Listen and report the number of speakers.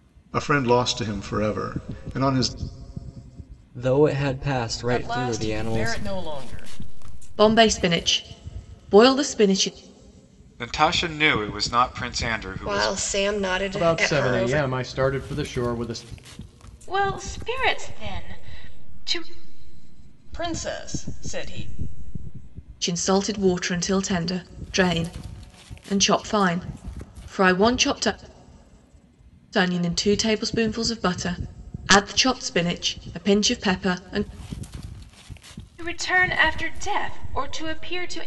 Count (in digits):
8